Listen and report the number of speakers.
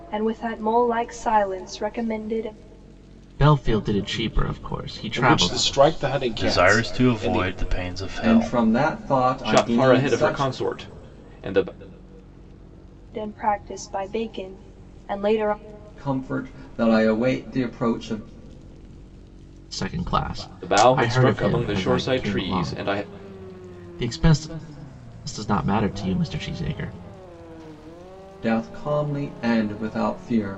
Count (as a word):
six